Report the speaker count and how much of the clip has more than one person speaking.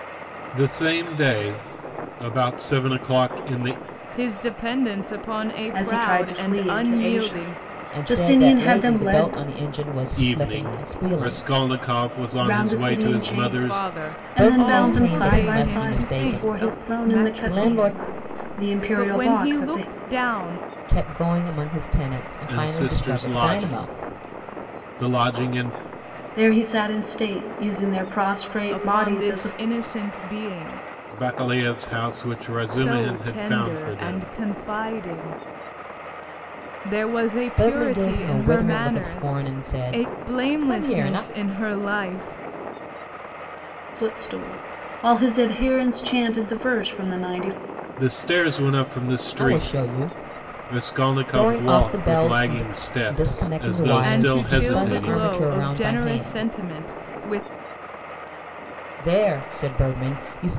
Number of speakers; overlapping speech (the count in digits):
4, about 44%